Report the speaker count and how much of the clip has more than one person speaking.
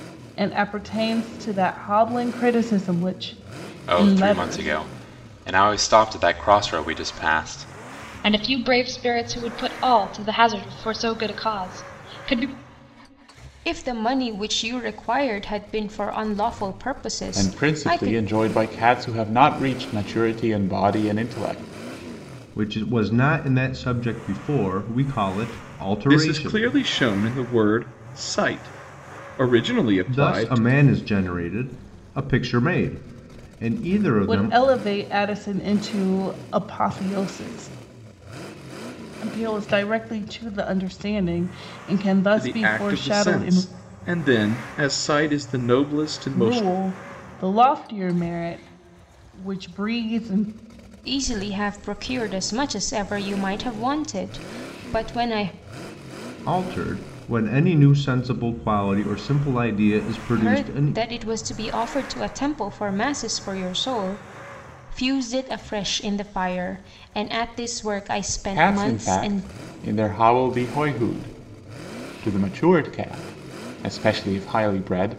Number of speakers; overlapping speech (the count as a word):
seven, about 9%